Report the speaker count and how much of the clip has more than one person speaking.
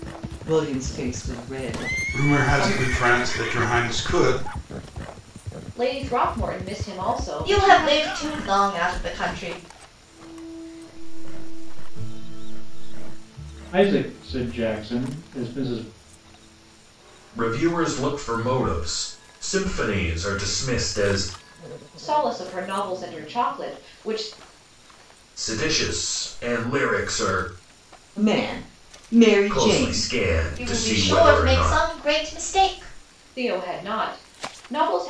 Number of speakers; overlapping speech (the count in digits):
7, about 10%